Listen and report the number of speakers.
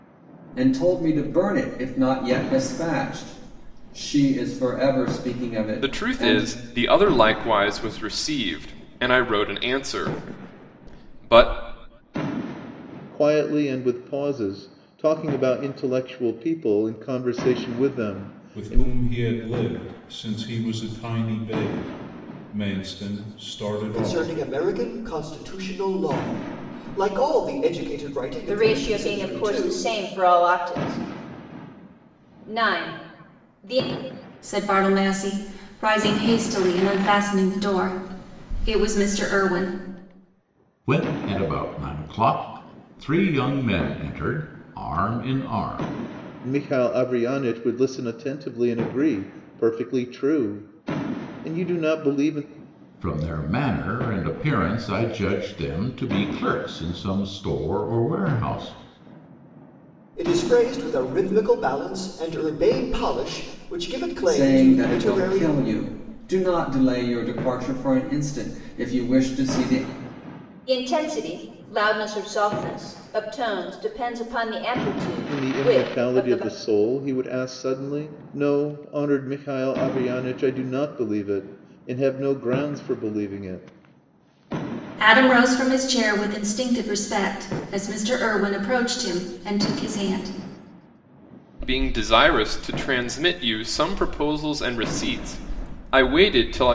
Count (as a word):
eight